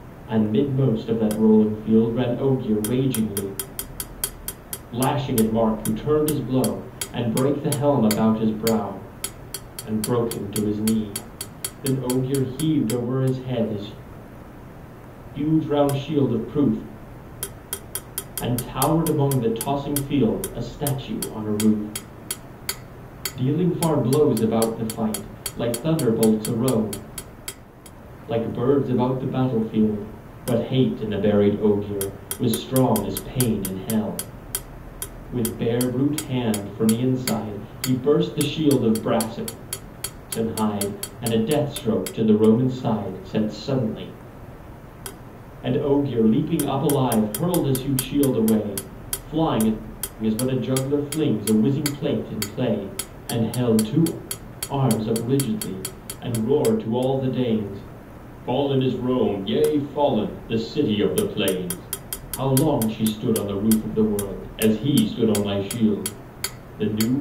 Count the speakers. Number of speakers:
one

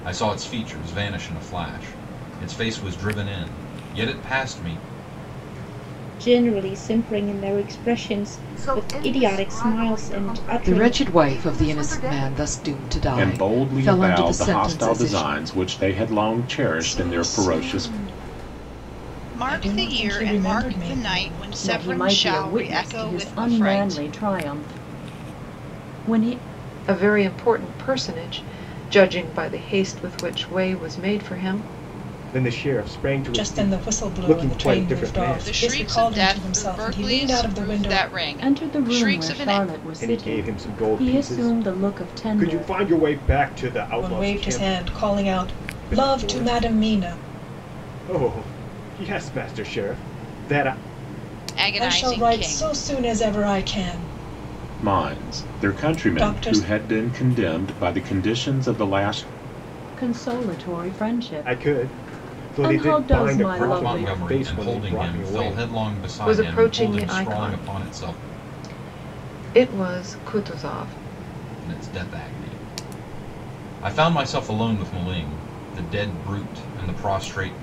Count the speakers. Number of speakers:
ten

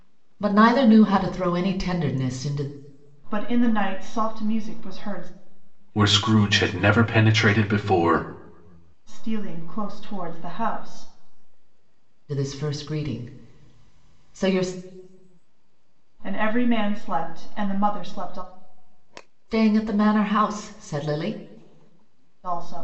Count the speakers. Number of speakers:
three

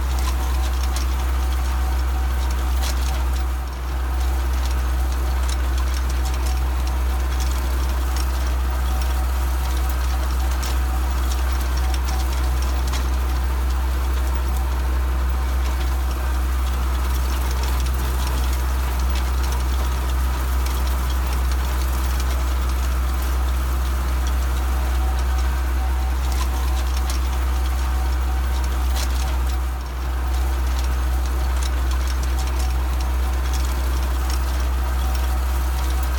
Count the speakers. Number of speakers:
zero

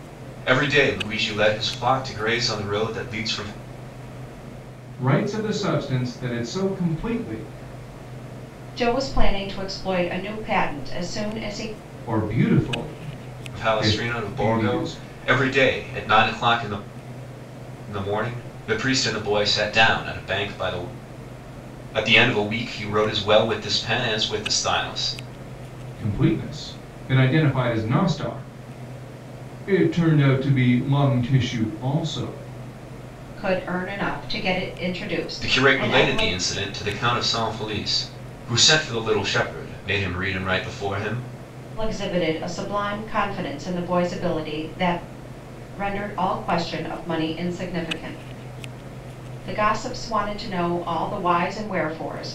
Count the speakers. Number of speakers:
three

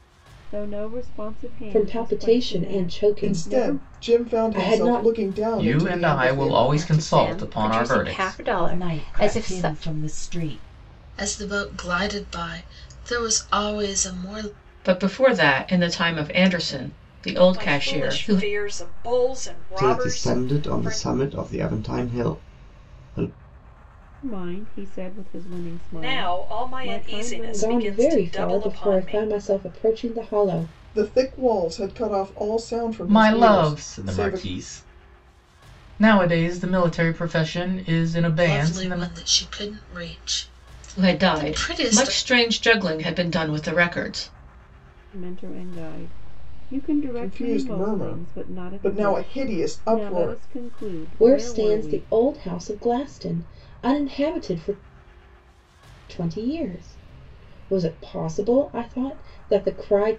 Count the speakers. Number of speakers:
ten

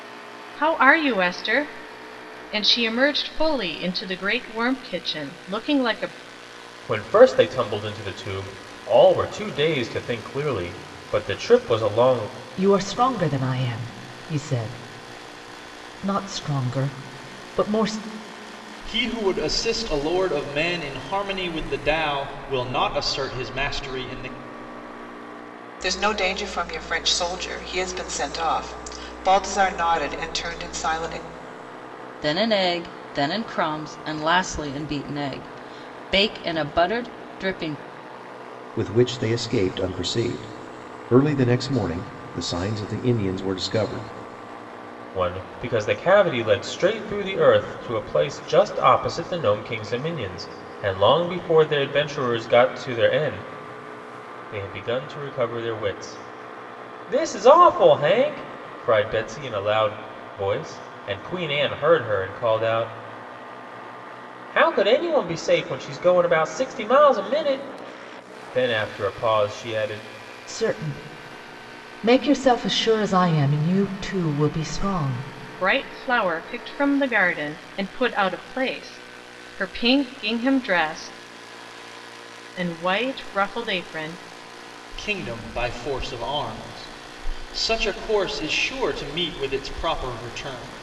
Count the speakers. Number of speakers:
seven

